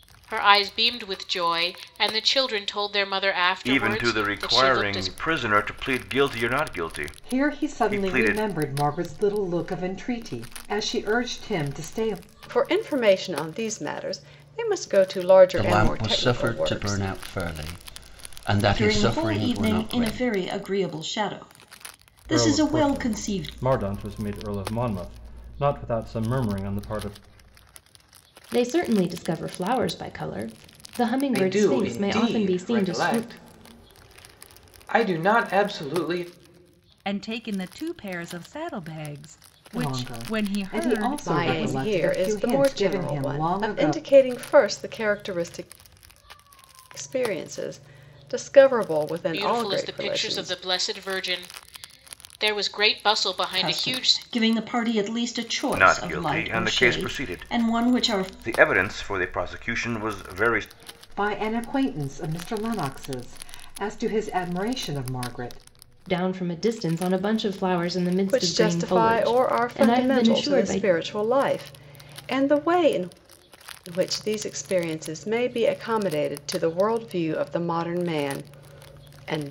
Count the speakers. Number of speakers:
10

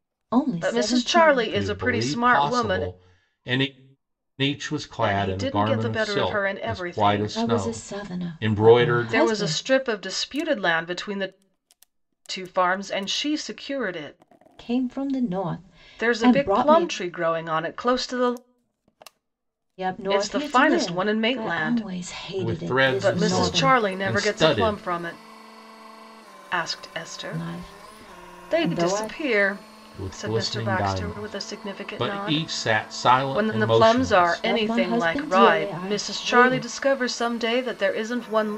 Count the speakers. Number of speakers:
3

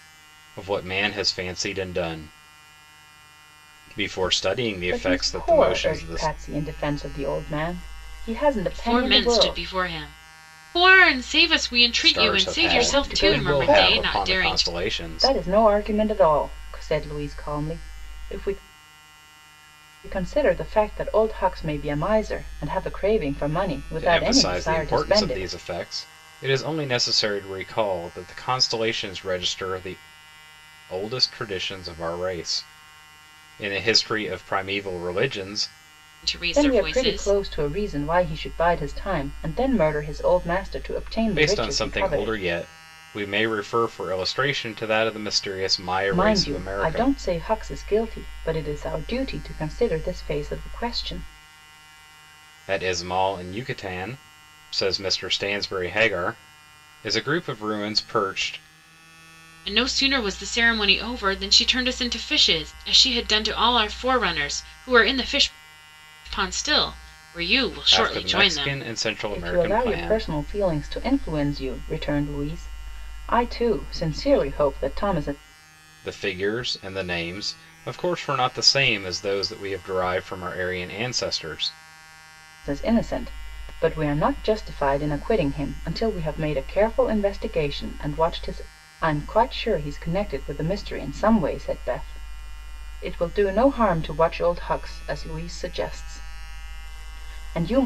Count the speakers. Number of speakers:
3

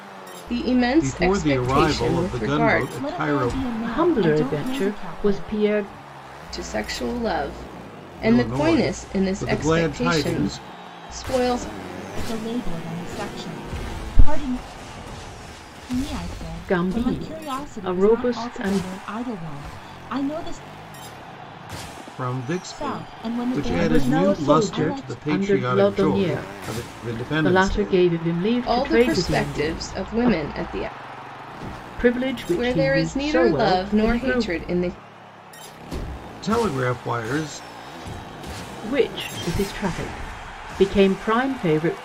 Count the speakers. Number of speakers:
4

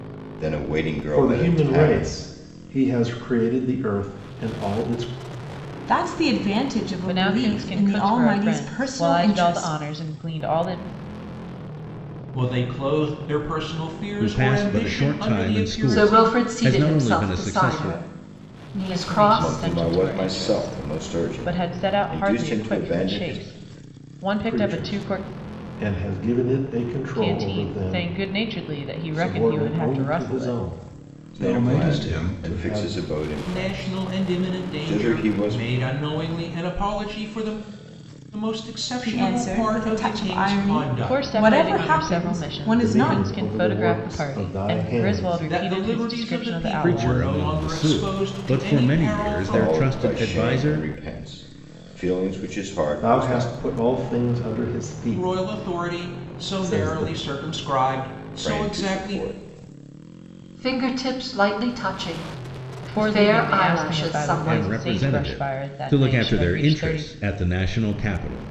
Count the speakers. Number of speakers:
7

